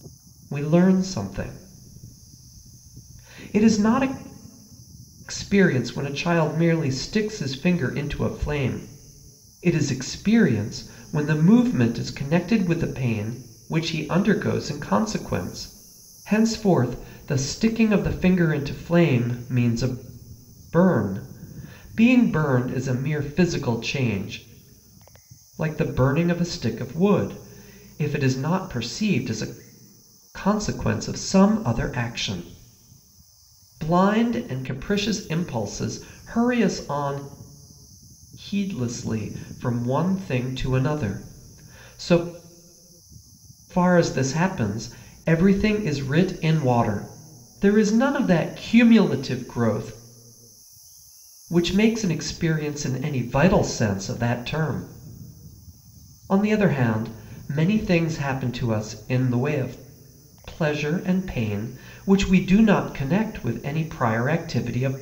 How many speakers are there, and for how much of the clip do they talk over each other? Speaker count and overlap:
1, no overlap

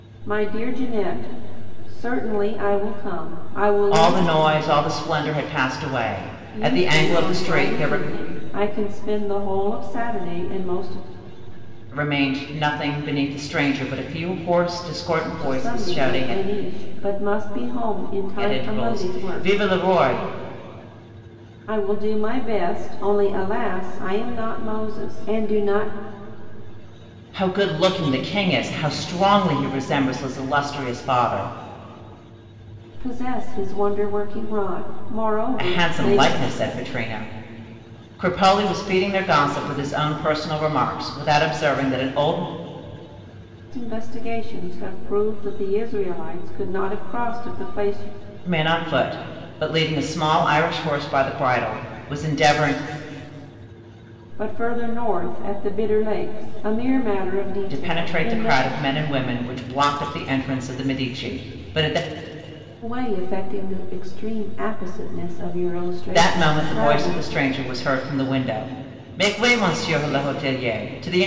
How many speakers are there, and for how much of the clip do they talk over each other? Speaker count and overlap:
2, about 10%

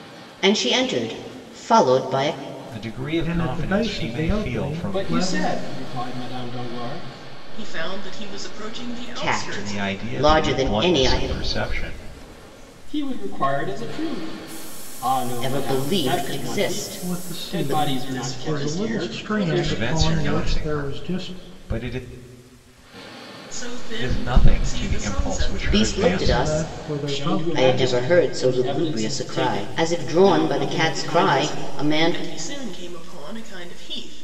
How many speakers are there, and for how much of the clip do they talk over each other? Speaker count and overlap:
5, about 53%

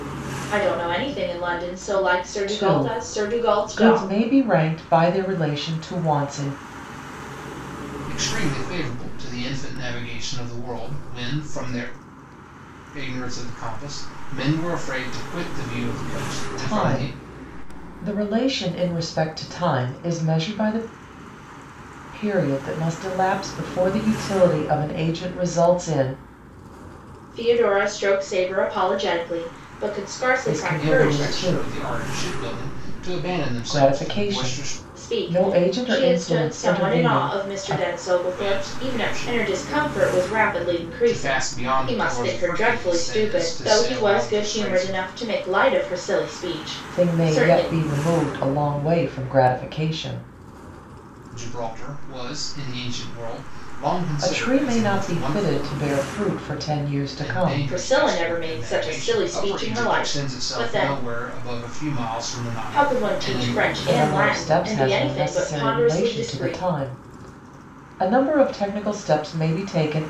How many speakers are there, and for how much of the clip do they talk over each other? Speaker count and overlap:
3, about 32%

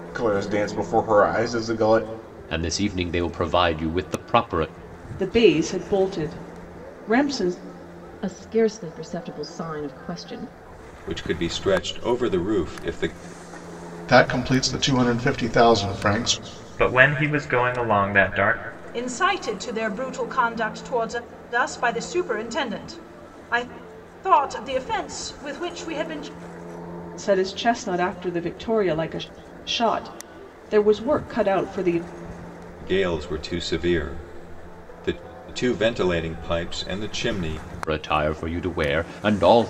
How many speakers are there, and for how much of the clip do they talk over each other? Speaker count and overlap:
8, no overlap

